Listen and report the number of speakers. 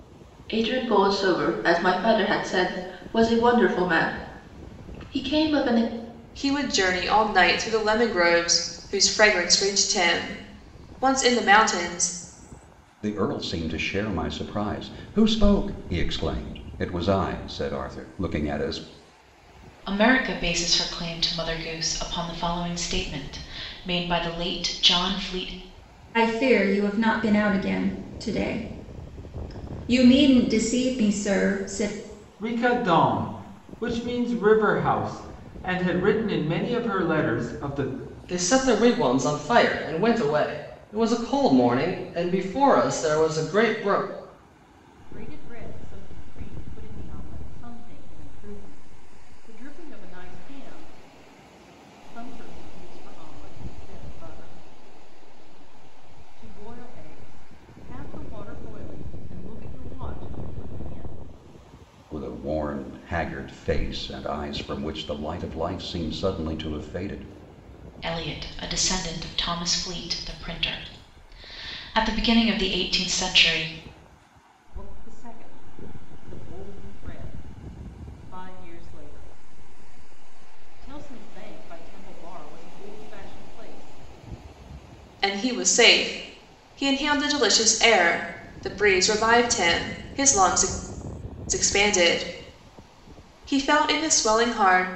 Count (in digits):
8